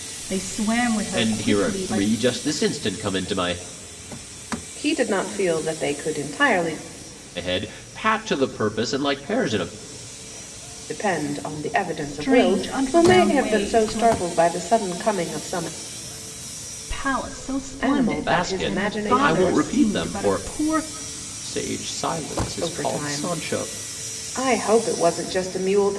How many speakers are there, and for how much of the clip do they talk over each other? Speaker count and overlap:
3, about 26%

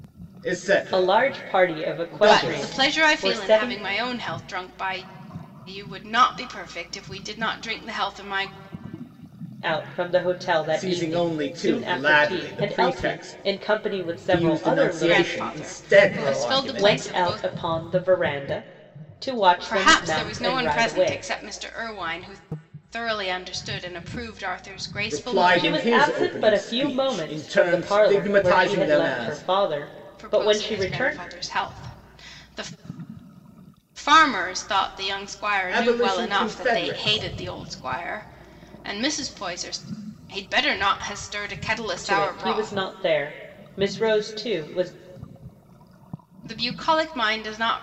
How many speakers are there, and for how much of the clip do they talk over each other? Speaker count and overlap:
3, about 39%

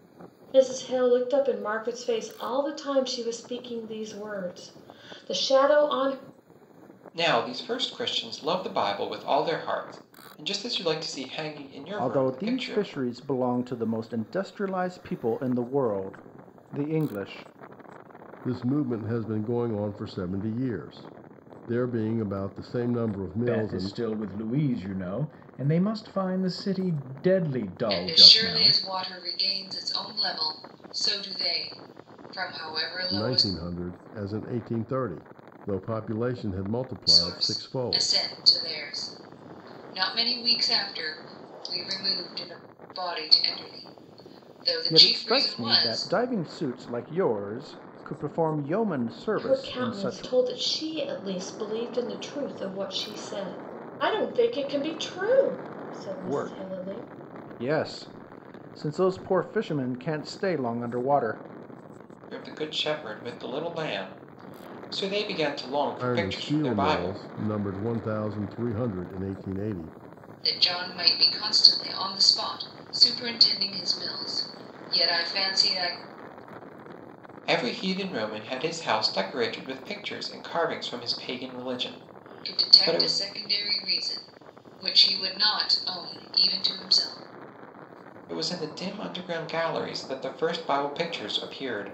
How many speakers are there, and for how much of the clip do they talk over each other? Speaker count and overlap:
6, about 10%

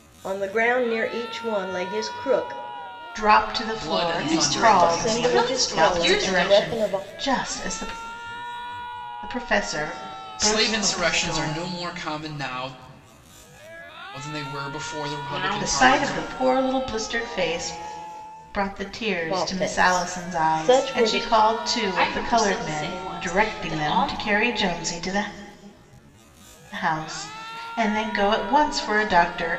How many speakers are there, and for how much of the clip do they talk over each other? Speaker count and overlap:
4, about 33%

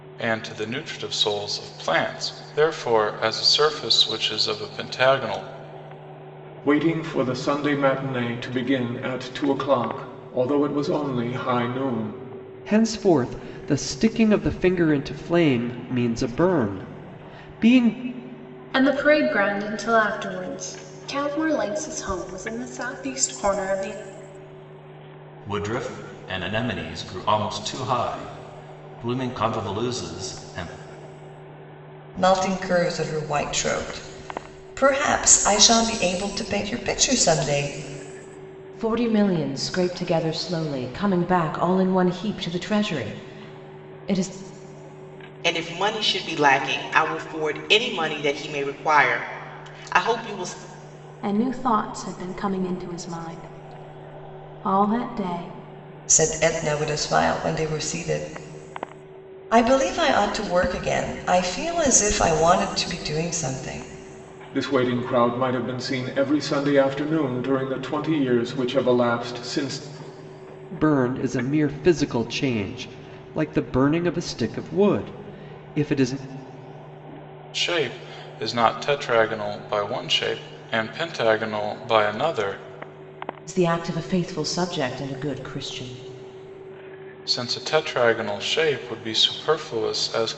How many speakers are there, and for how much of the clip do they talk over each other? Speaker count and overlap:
9, no overlap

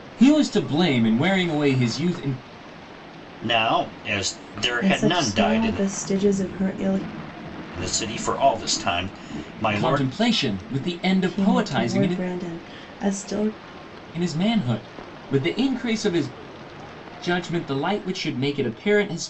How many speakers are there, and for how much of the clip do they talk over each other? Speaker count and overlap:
3, about 13%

